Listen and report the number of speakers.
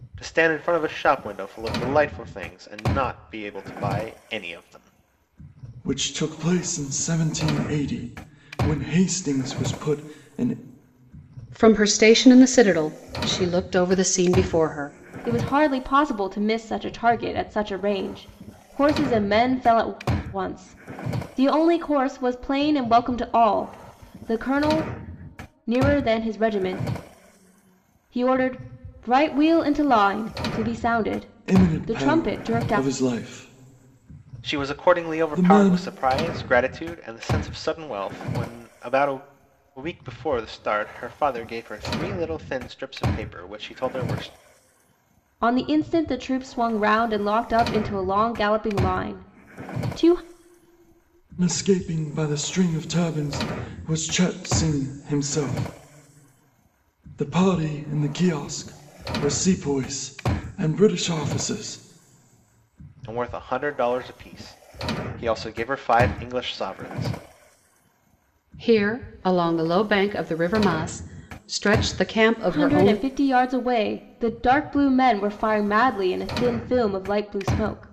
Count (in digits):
4